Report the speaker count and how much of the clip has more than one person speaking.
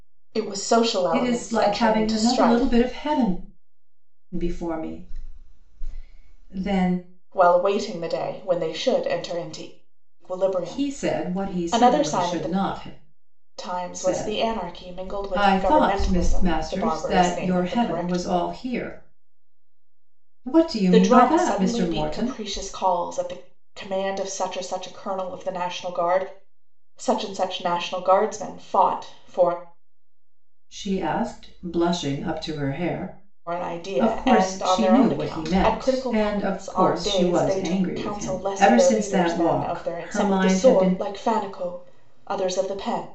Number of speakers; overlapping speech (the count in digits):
2, about 38%